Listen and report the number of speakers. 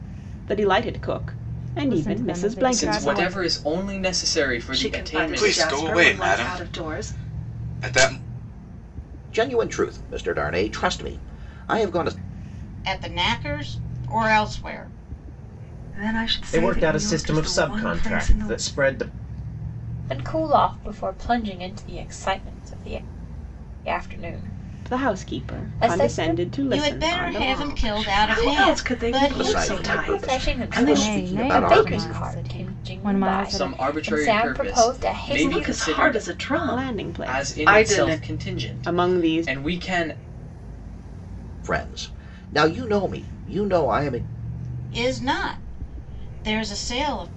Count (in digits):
10